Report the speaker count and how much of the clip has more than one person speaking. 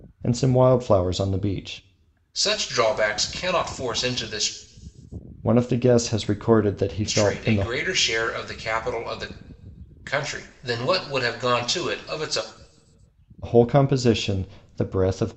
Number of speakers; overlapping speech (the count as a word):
two, about 4%